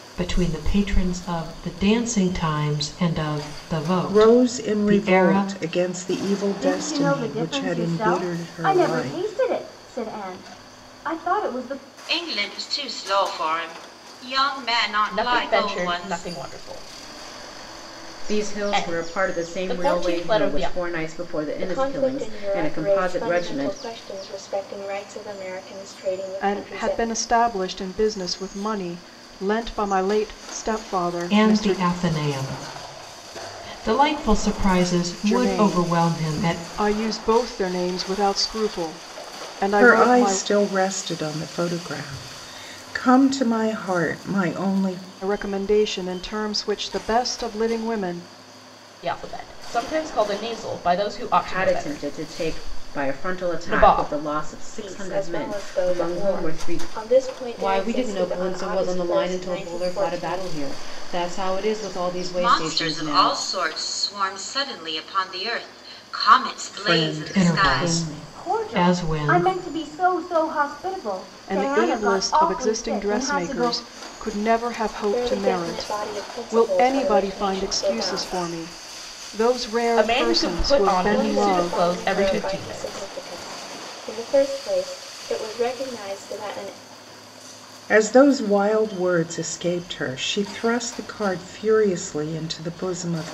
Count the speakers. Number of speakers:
eight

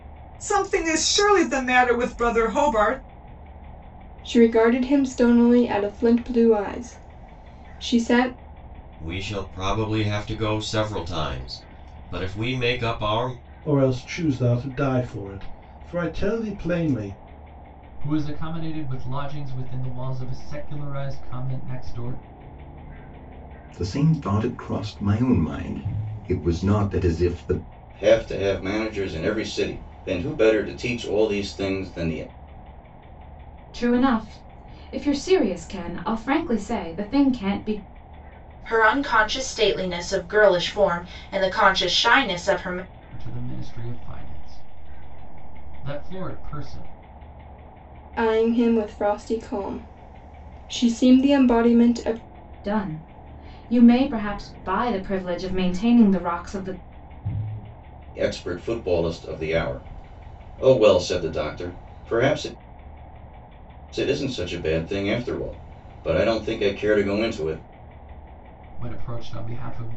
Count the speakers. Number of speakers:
nine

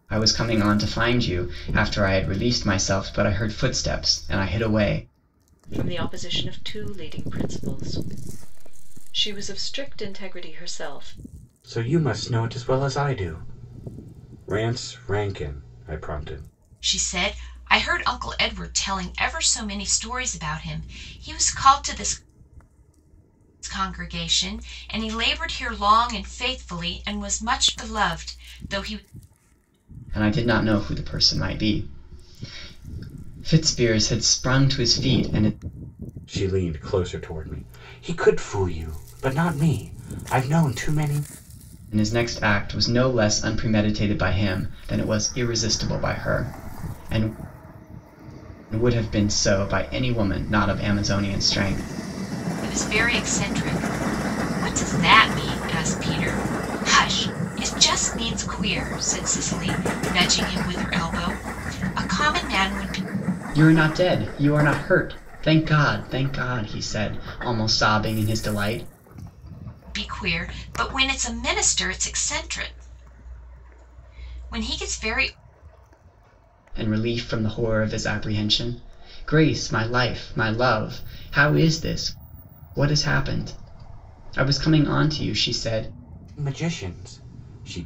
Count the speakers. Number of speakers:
four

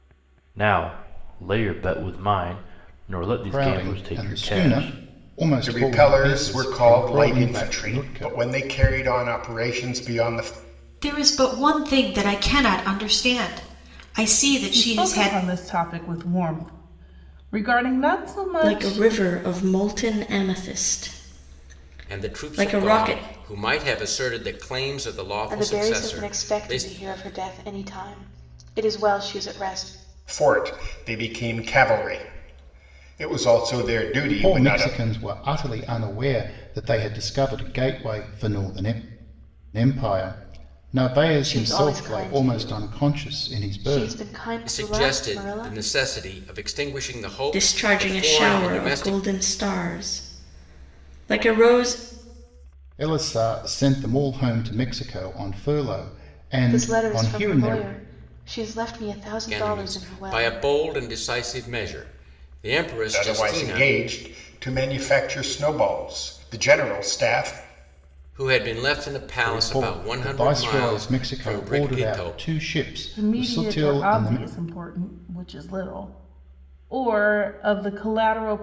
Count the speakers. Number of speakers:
eight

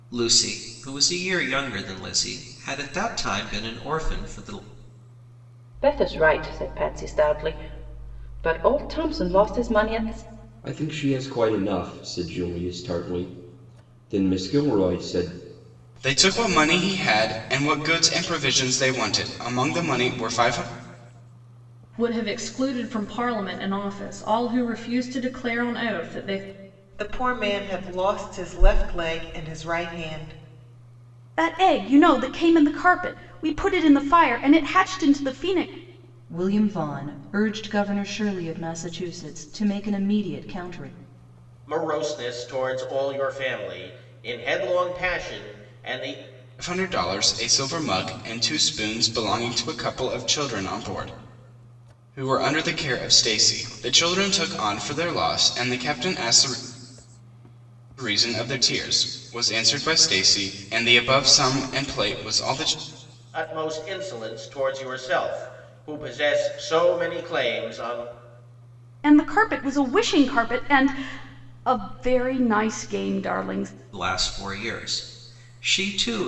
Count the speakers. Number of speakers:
nine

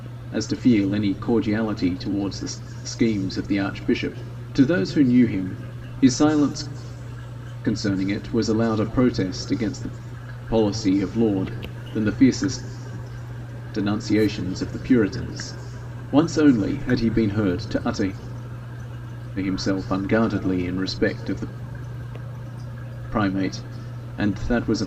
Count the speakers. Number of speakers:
one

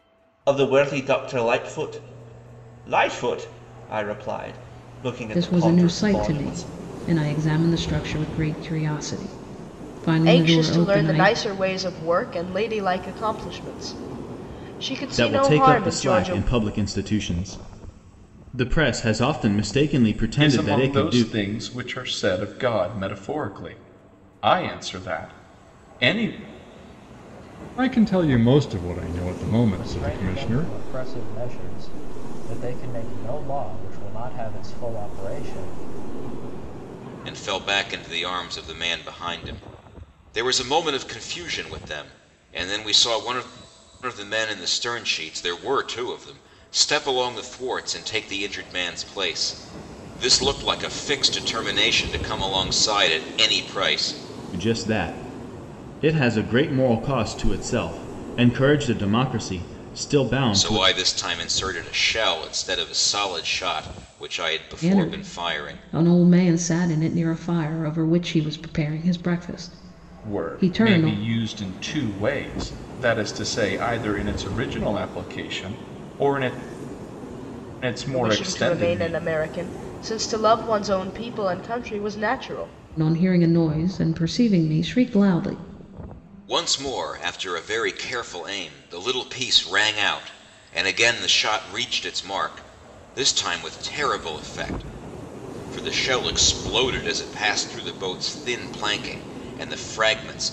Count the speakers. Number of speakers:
eight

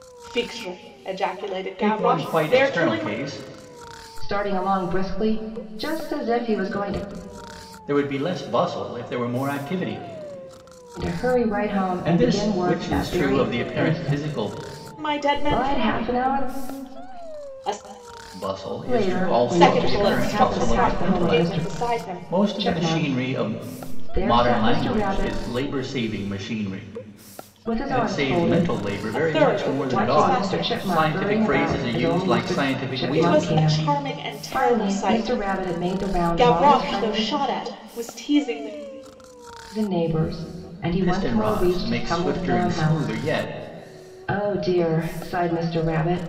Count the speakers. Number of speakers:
three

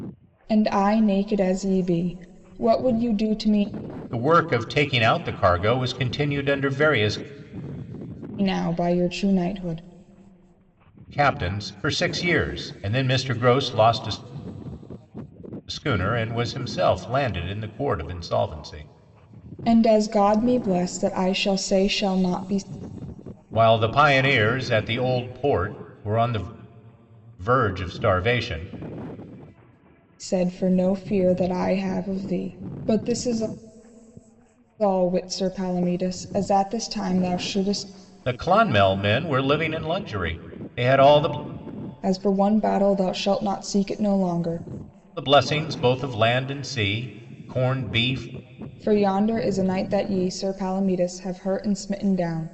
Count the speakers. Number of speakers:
two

